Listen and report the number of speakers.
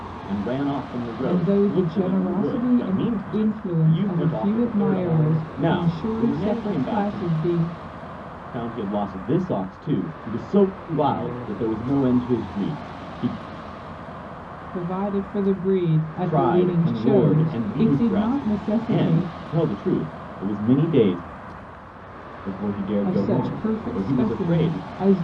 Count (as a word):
two